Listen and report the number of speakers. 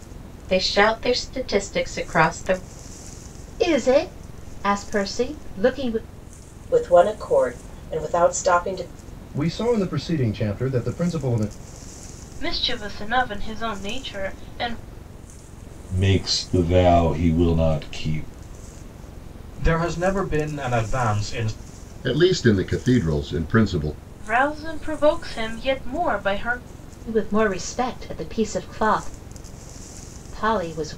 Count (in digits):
8